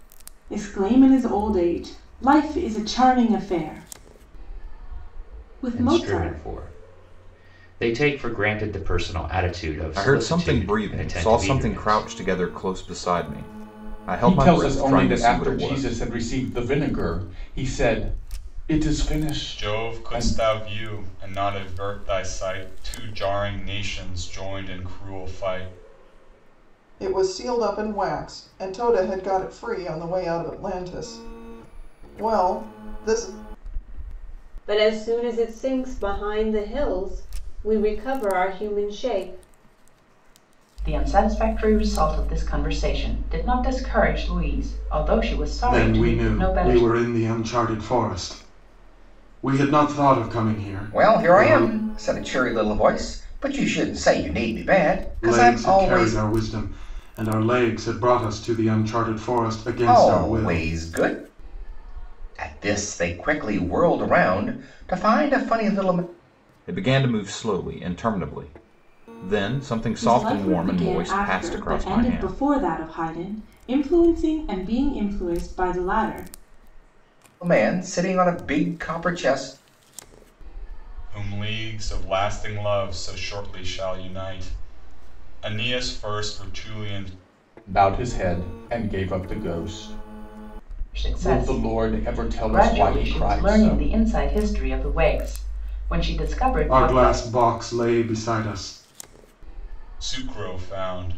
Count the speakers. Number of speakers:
10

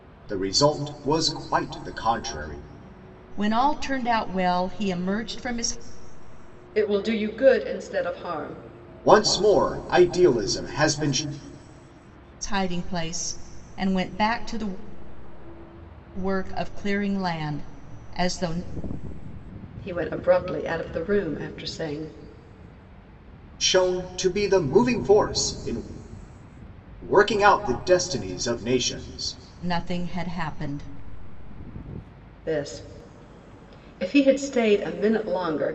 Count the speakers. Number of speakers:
3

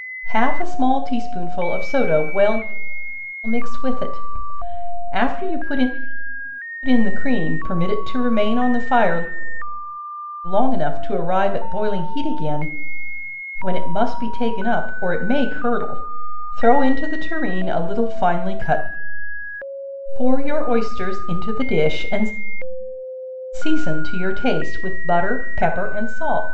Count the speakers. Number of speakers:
1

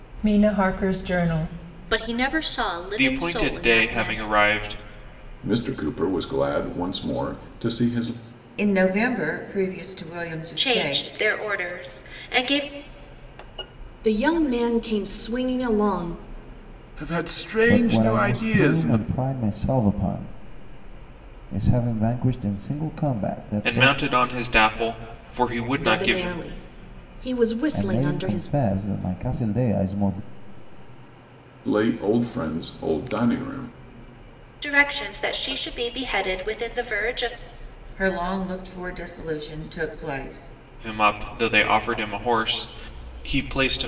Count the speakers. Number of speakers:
9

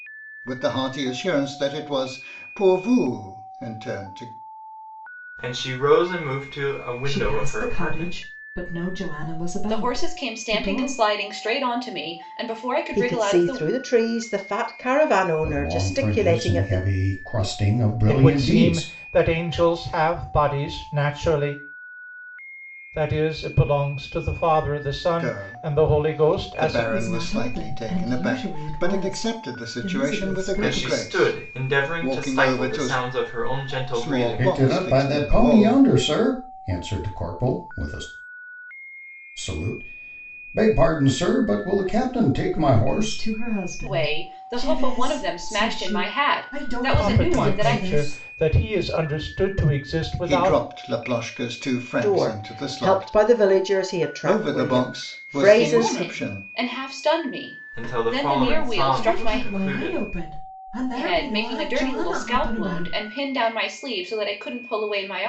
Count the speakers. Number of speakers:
7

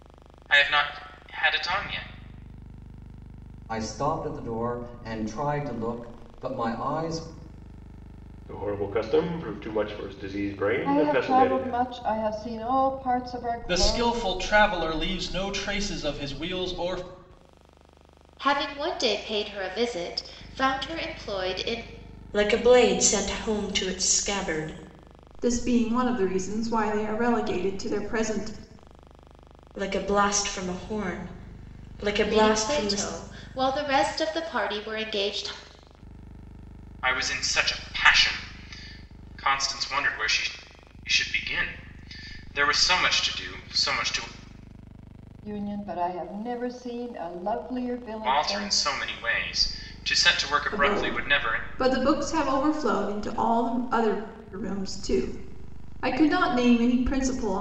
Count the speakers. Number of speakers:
8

